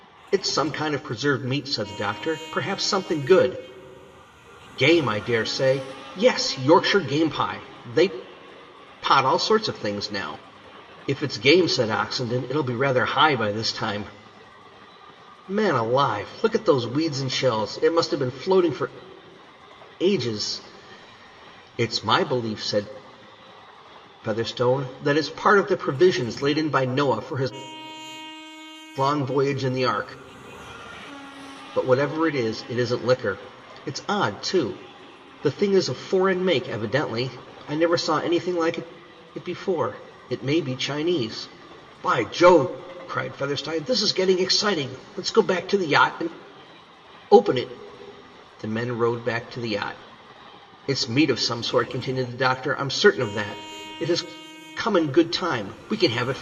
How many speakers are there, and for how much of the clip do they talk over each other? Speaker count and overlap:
1, no overlap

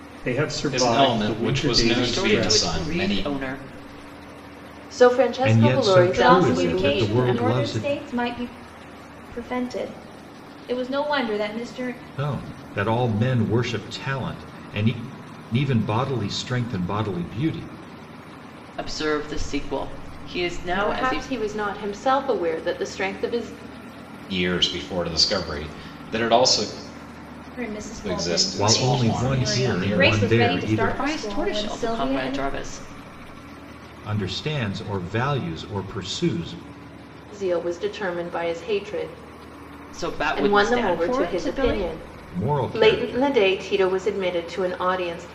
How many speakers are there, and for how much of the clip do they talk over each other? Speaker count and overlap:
6, about 28%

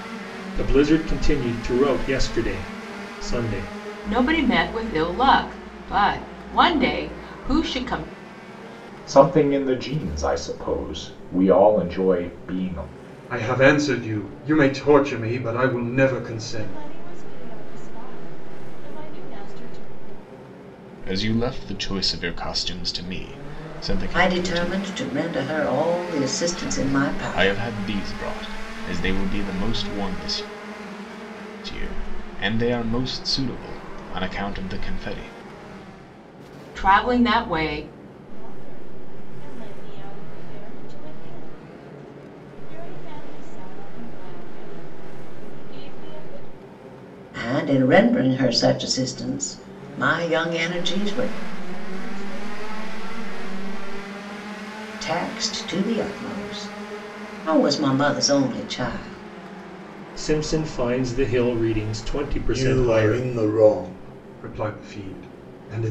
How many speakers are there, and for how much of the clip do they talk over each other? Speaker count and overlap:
7, about 5%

